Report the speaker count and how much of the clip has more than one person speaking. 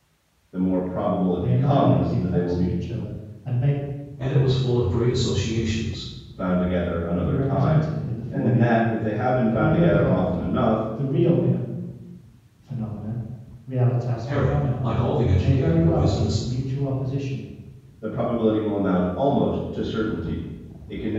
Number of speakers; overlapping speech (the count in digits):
3, about 30%